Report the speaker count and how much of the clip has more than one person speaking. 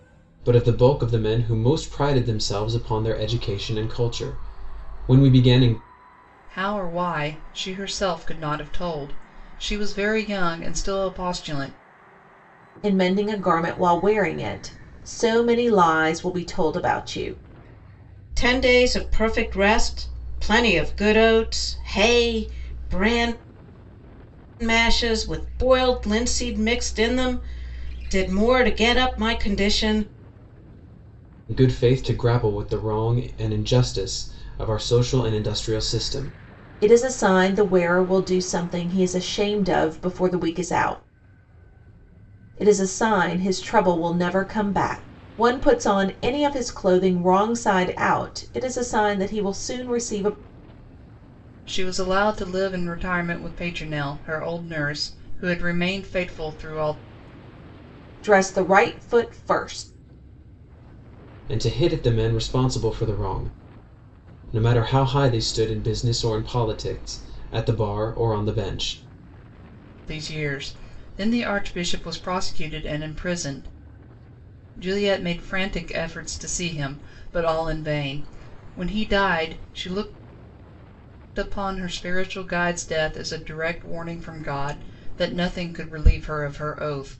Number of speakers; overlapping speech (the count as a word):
four, no overlap